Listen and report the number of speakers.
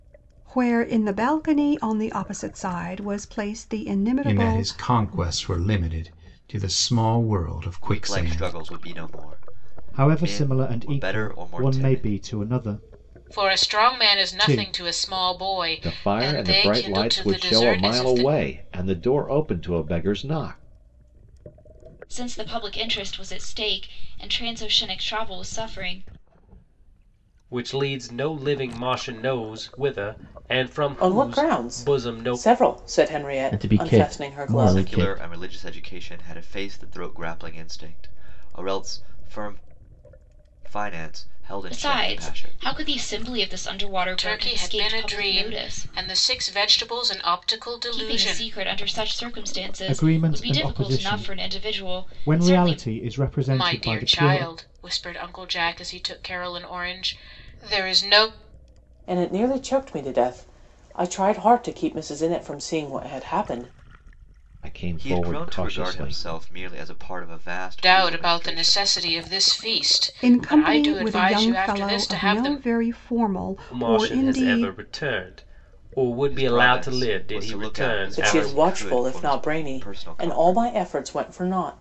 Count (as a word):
ten